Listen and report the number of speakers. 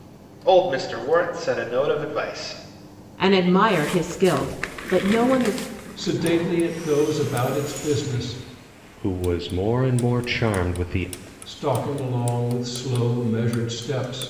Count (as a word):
four